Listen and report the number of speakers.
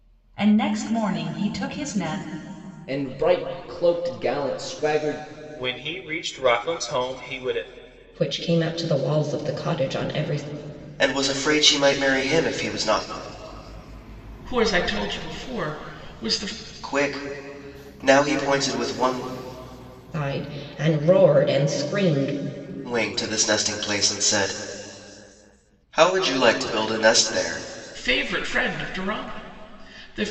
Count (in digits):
6